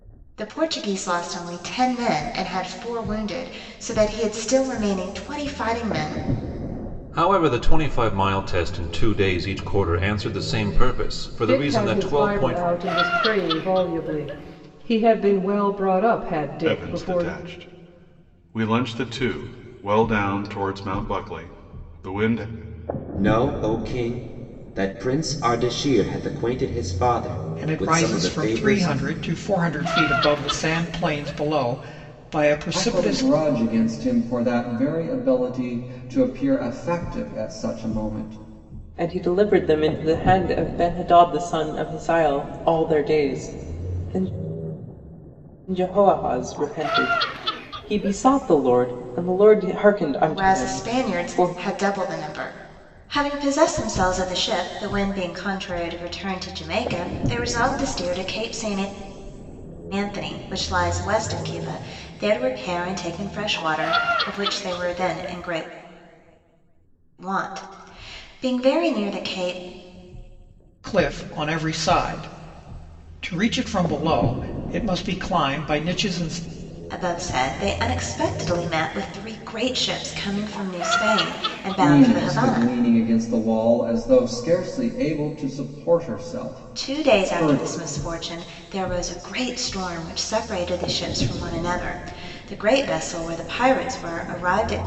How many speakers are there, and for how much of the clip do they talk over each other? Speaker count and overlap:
8, about 7%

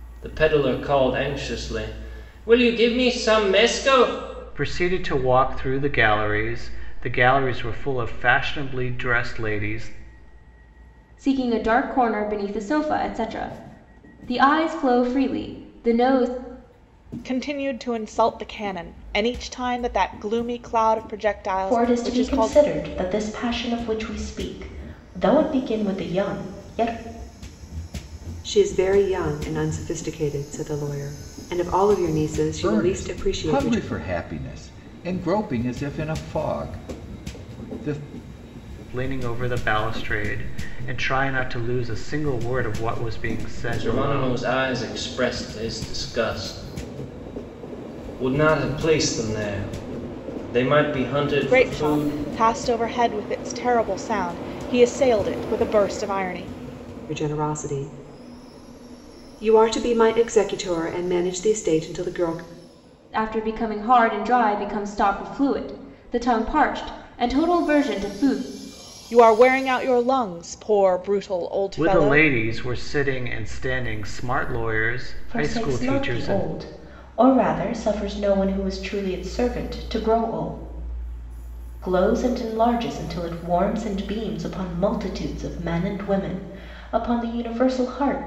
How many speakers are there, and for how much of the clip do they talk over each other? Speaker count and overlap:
7, about 6%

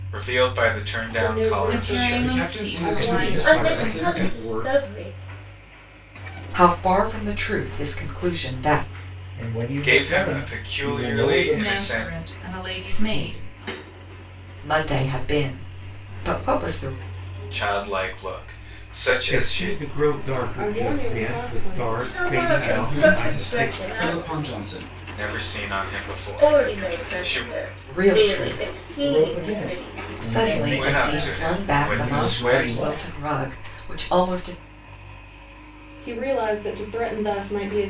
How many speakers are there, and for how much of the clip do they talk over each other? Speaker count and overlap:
8, about 45%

